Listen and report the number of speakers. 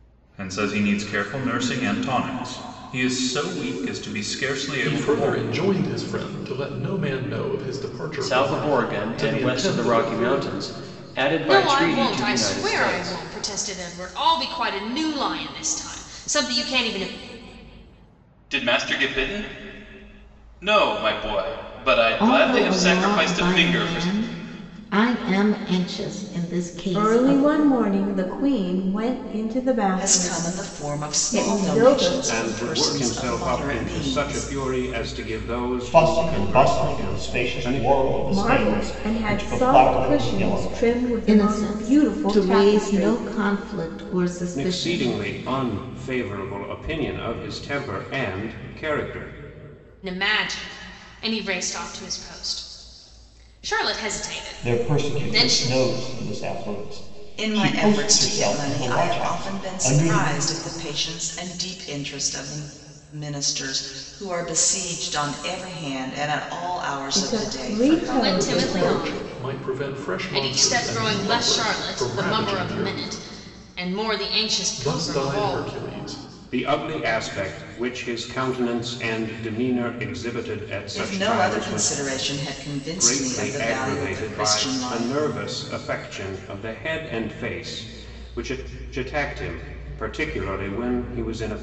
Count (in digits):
10